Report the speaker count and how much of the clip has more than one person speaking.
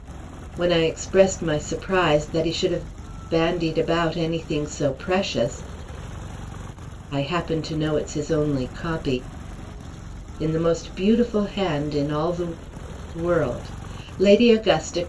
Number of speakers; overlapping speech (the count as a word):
one, no overlap